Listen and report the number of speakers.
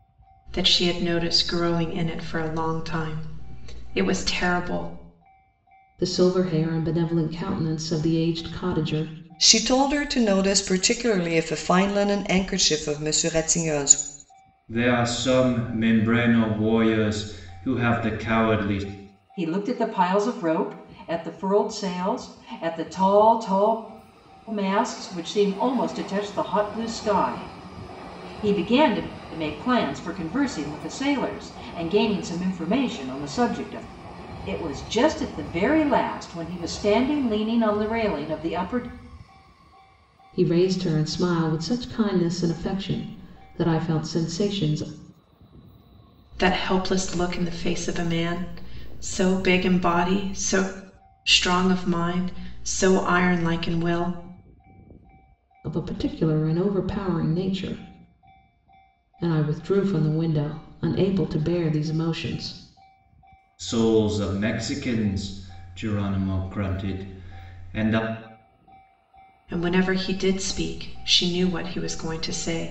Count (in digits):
5